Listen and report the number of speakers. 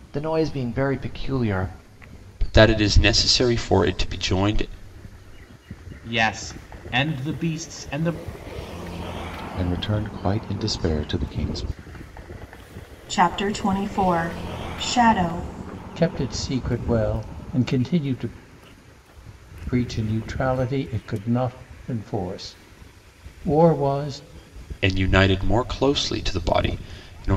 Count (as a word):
six